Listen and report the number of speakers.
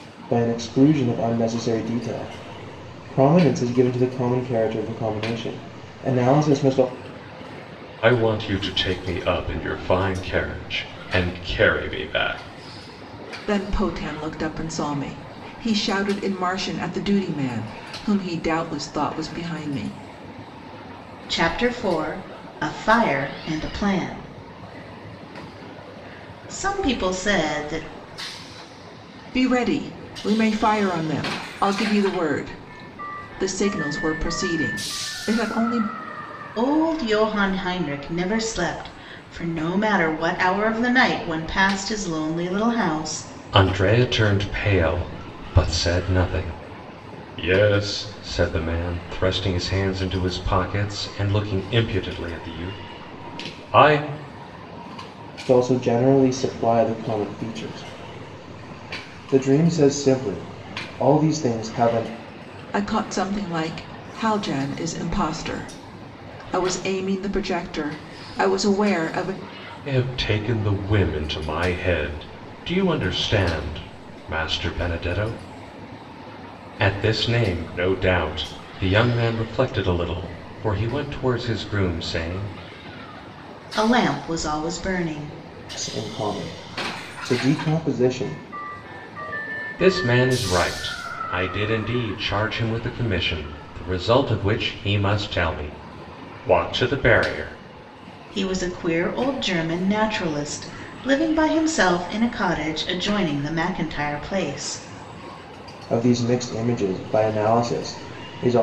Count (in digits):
4